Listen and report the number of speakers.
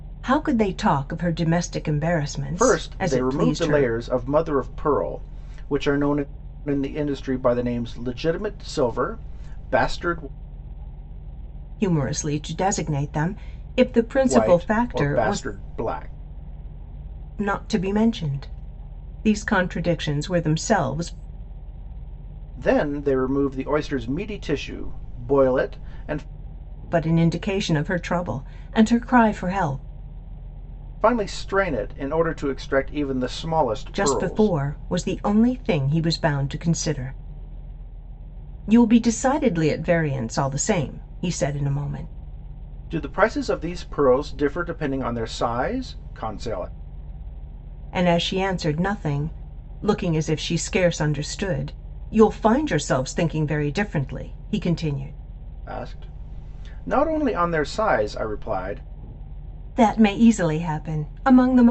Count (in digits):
2